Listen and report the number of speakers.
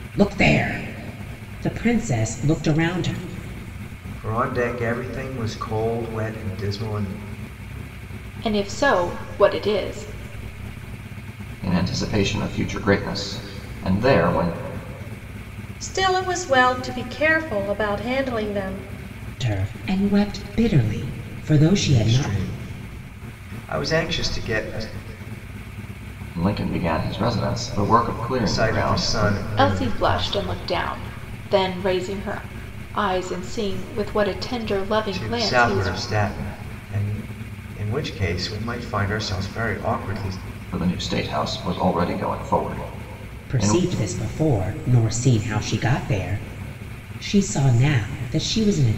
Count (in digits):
5